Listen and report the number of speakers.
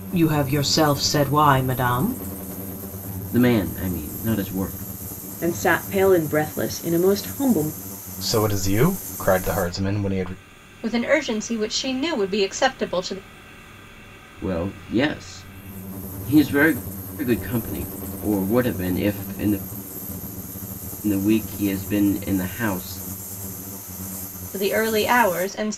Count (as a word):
five